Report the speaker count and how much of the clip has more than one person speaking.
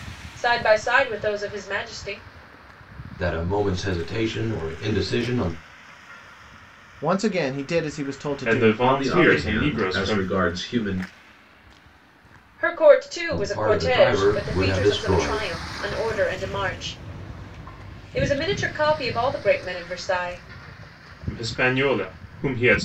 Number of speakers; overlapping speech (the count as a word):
five, about 18%